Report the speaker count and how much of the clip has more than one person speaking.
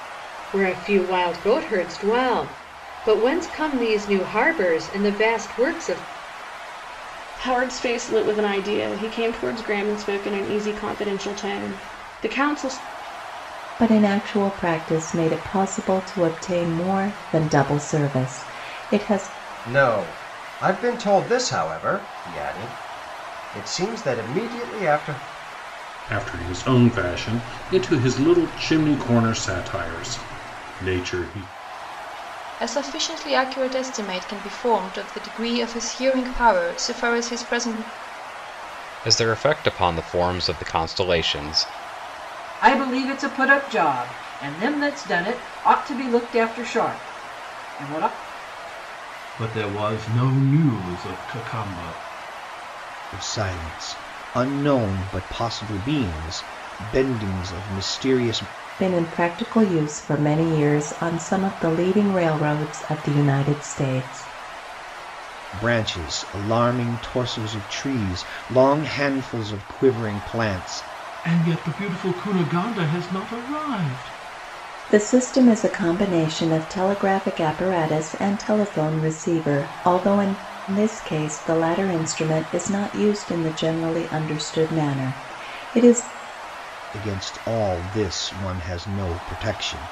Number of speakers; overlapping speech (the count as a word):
ten, no overlap